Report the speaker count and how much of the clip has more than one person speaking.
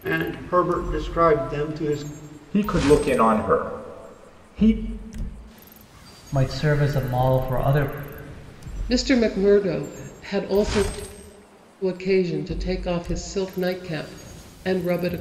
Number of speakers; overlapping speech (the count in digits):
4, no overlap